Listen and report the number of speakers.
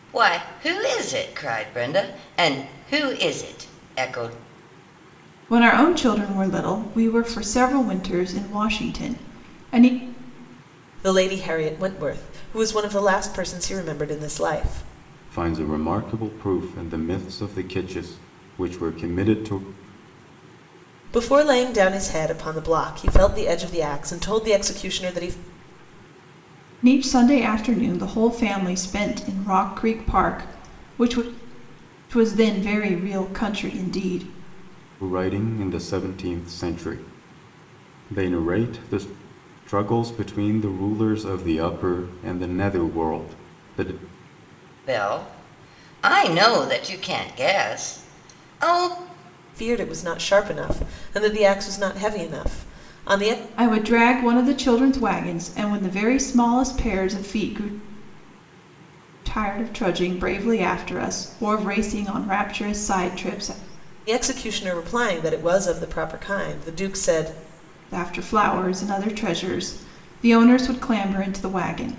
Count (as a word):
four